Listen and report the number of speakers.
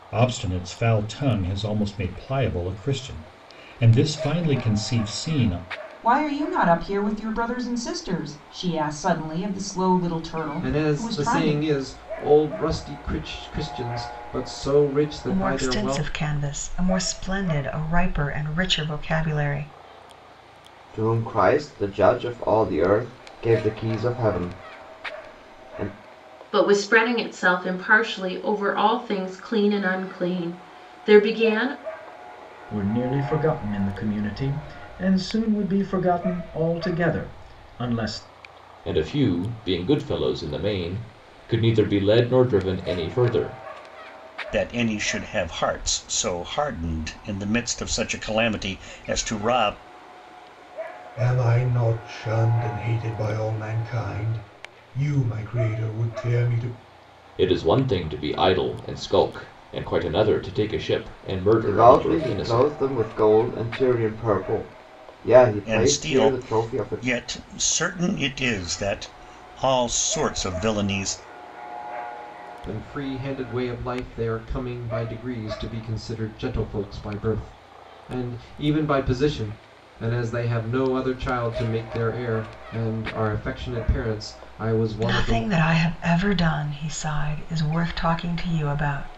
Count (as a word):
ten